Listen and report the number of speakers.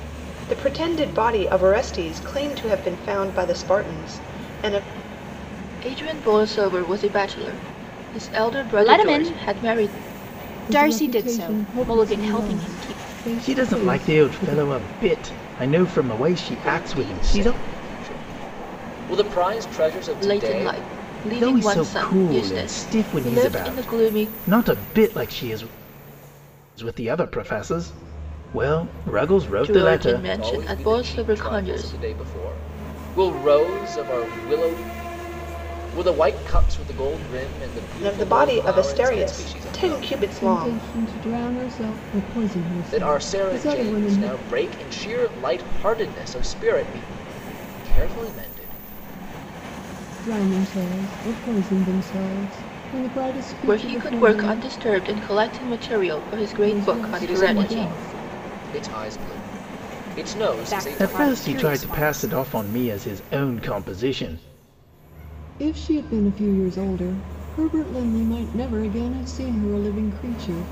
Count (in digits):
6